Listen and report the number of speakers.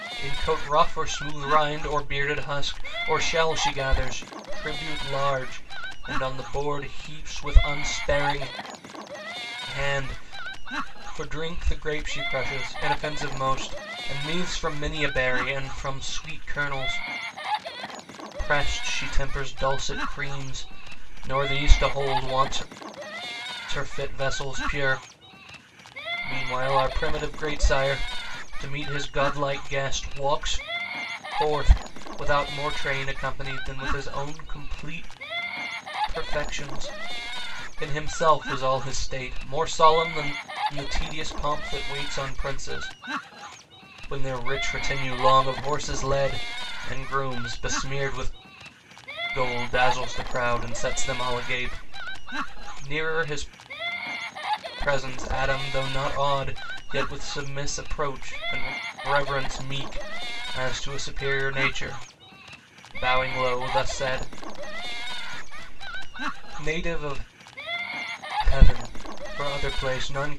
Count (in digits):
1